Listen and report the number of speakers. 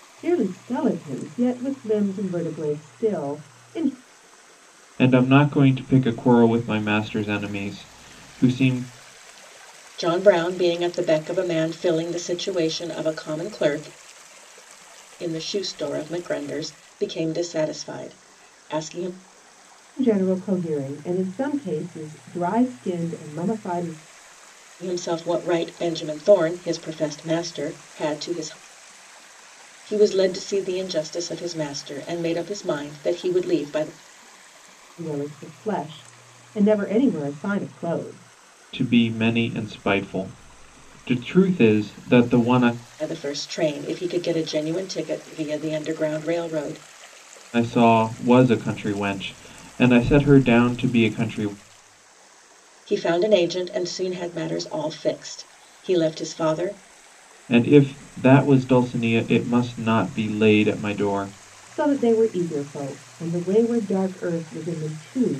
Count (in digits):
3